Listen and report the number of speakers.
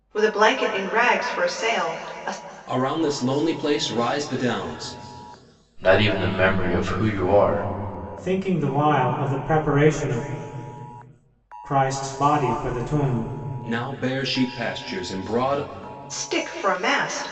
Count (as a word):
four